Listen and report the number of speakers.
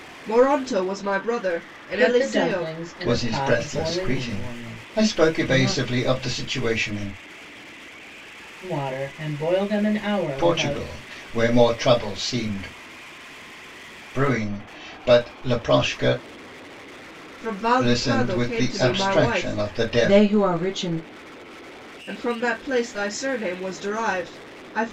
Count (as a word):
four